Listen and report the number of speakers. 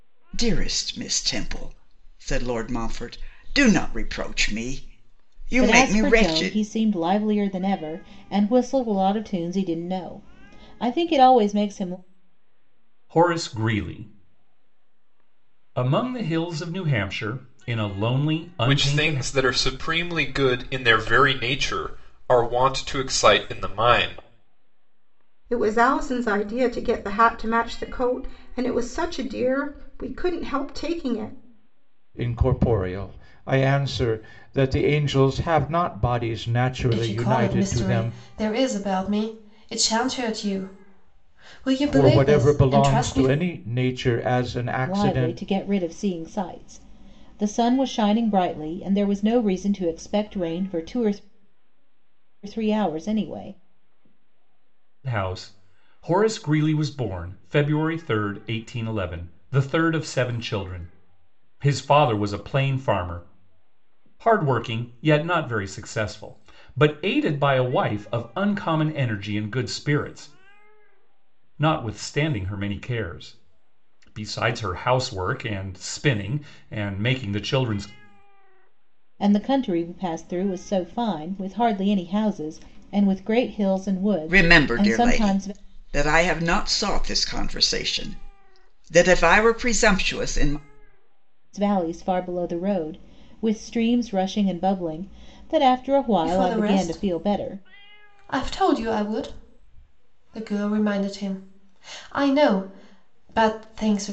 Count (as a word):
seven